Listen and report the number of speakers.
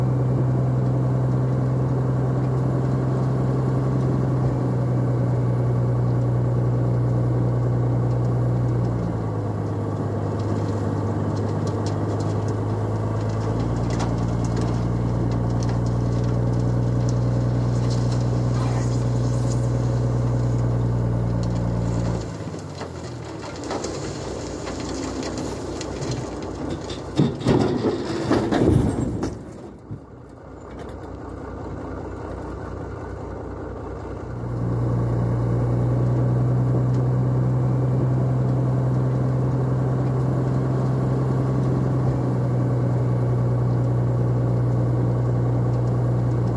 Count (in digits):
0